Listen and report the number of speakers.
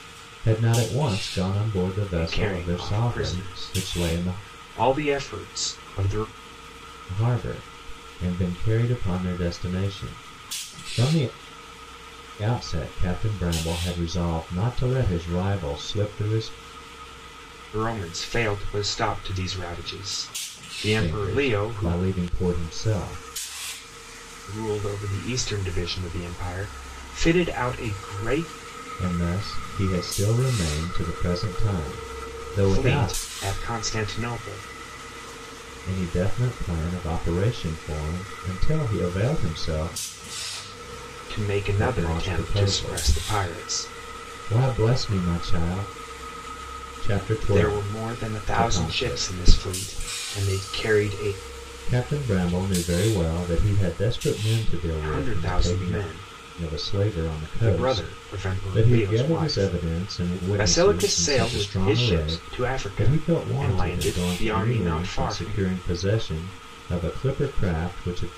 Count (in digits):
2